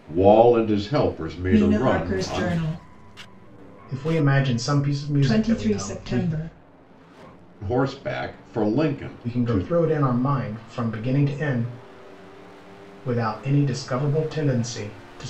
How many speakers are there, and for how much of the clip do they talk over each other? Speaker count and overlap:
3, about 17%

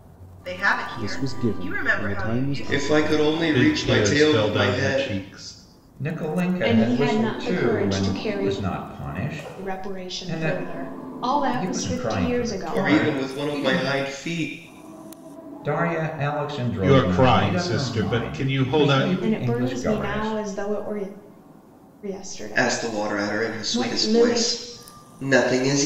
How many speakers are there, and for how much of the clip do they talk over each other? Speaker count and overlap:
6, about 58%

